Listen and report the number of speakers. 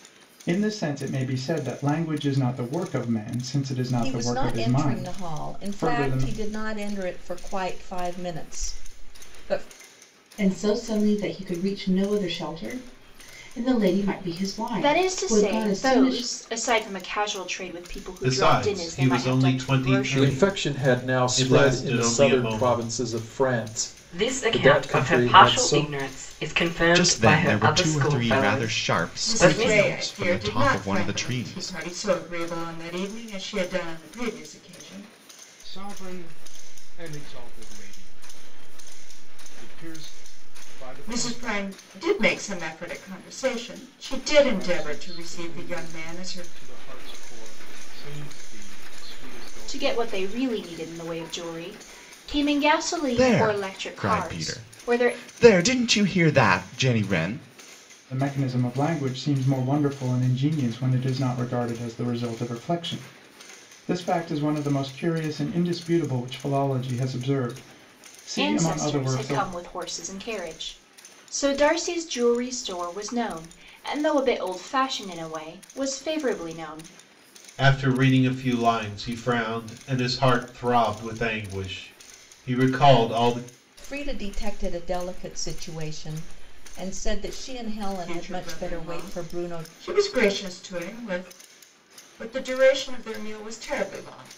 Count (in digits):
10